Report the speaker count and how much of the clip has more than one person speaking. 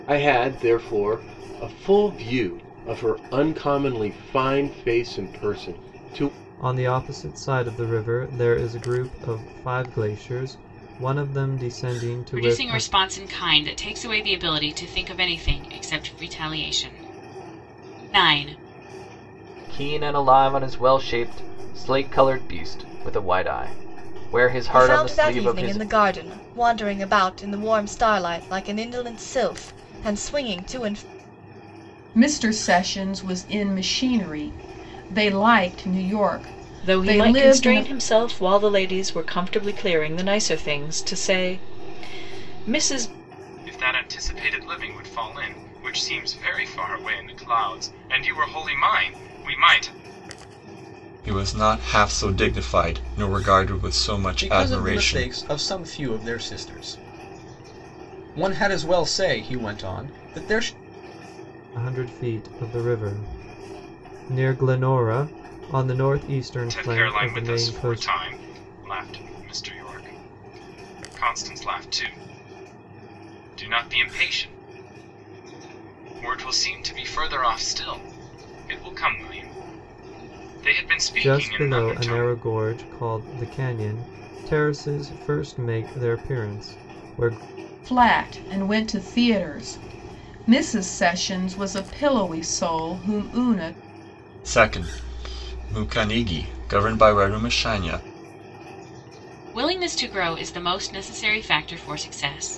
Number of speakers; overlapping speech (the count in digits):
10, about 6%